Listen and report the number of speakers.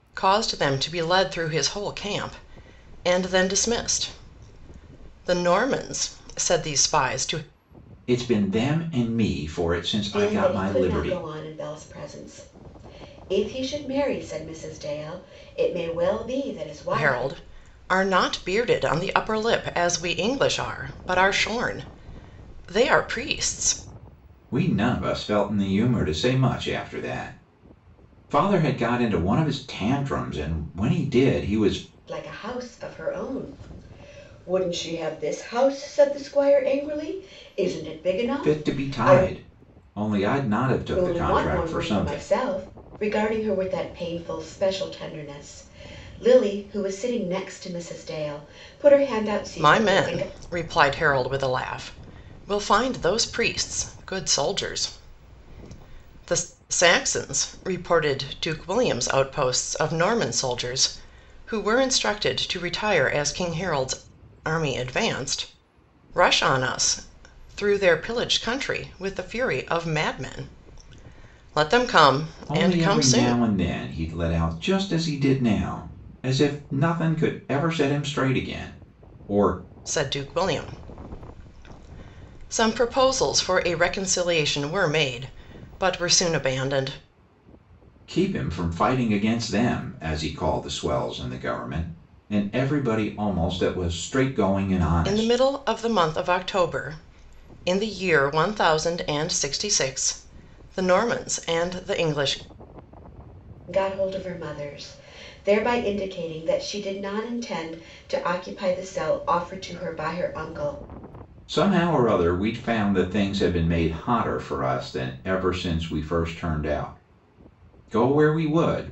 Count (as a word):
three